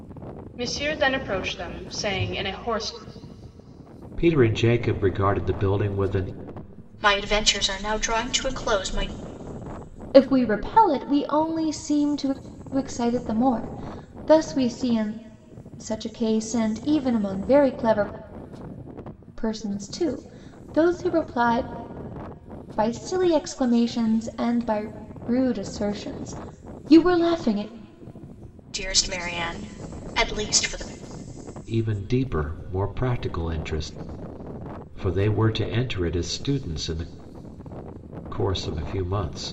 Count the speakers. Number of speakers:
4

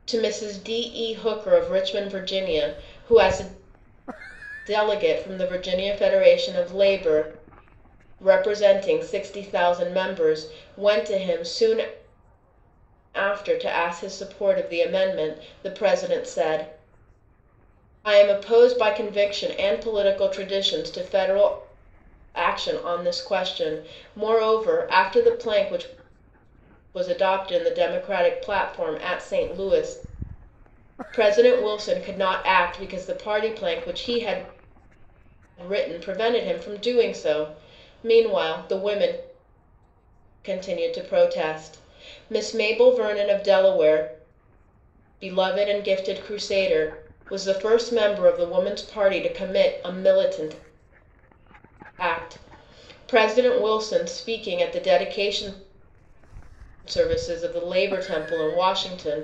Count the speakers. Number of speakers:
1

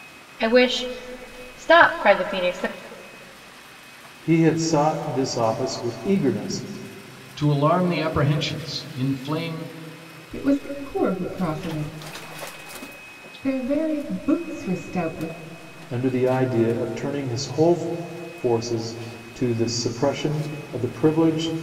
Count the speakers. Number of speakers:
4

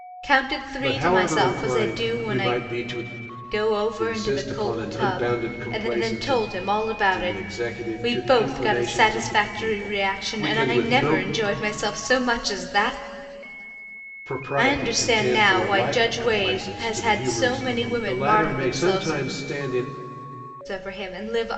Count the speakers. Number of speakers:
2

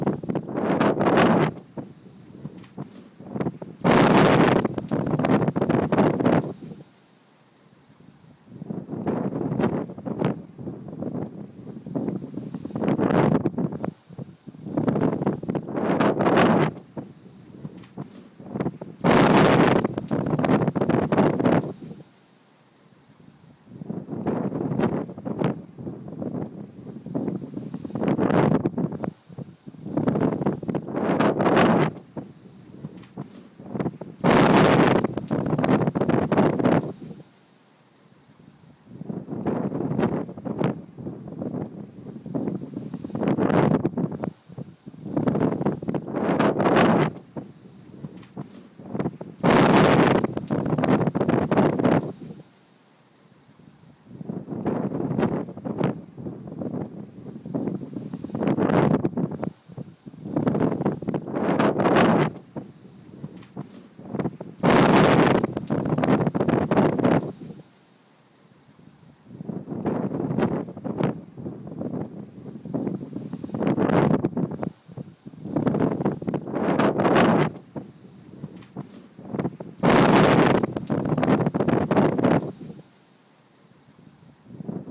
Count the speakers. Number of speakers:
0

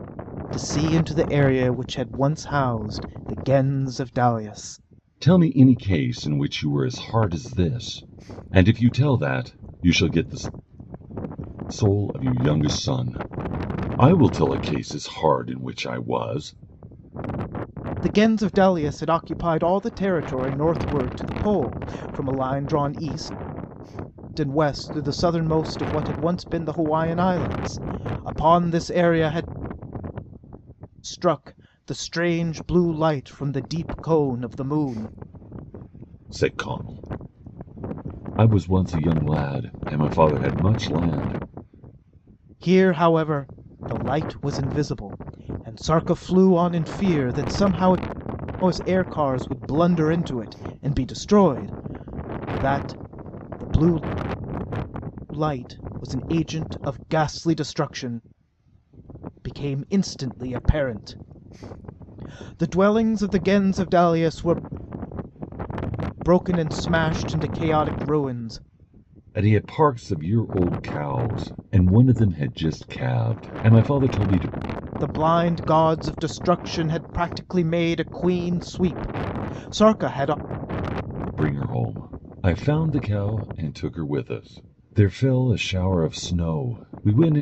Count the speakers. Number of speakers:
2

